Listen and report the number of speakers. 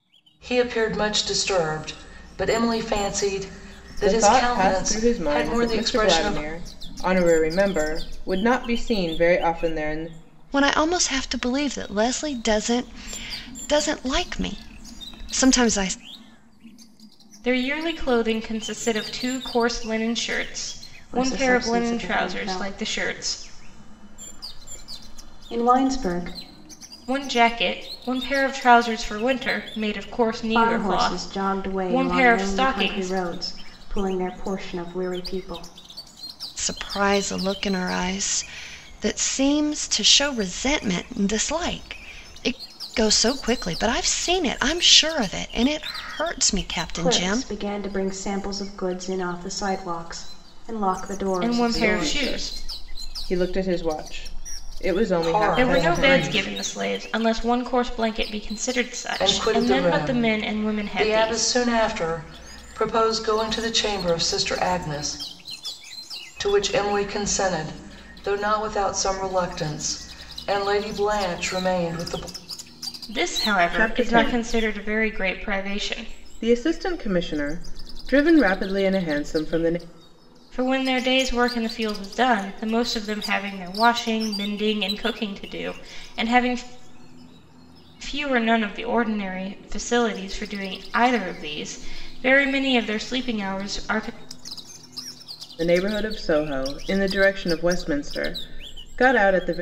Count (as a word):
five